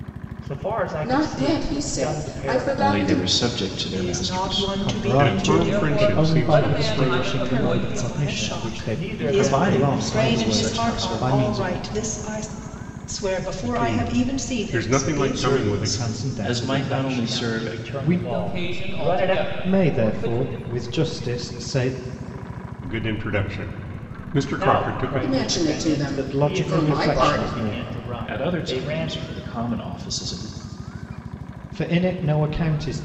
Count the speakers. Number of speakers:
seven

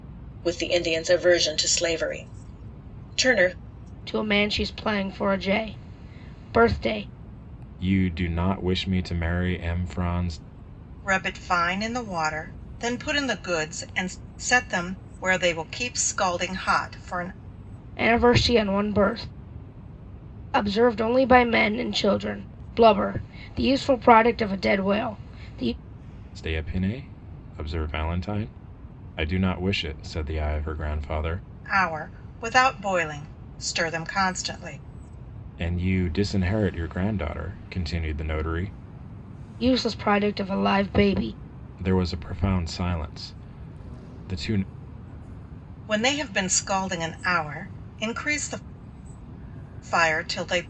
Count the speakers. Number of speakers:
four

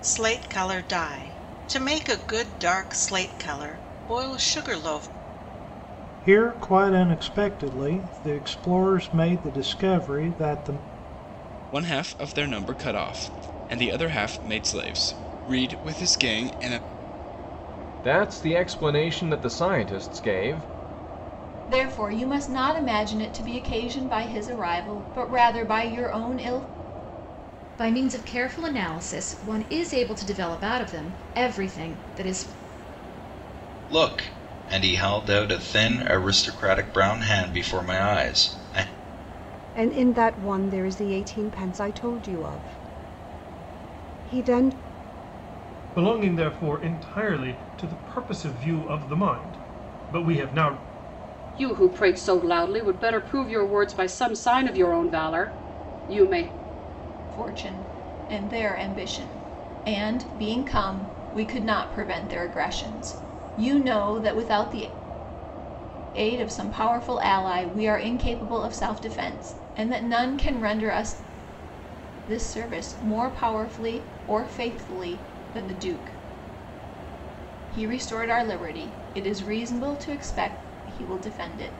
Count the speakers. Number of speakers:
ten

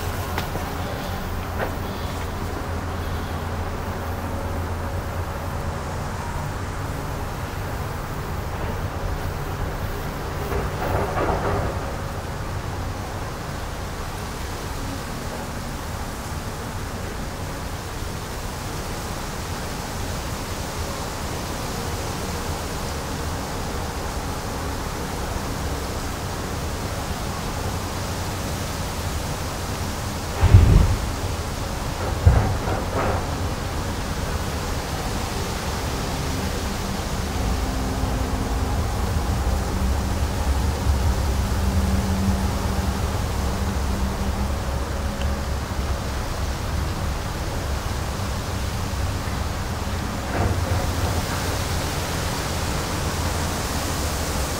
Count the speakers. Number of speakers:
zero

